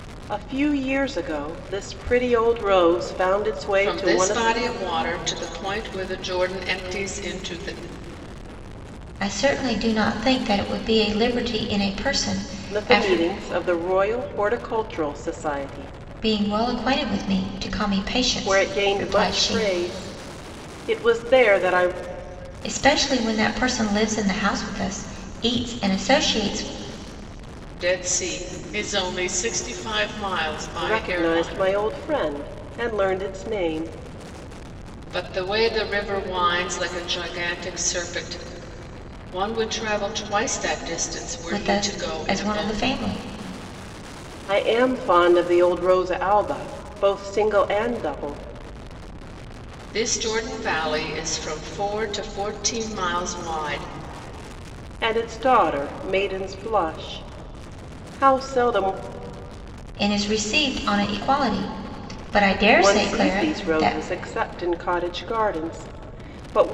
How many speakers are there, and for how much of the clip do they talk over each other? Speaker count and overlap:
three, about 9%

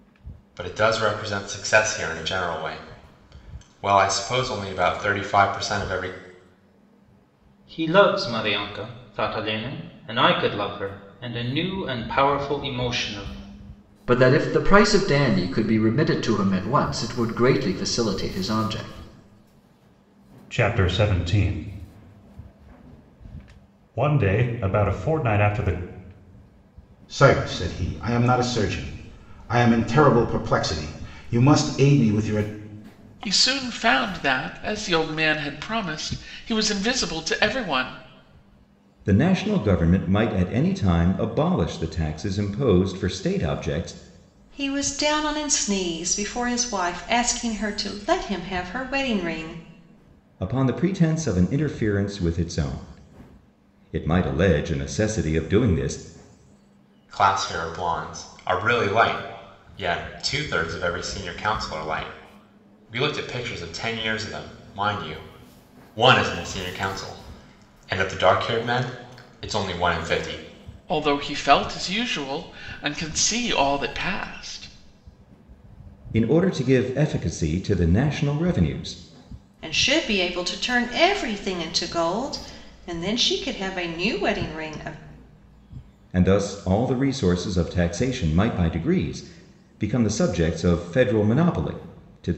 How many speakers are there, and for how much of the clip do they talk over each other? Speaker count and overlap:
eight, no overlap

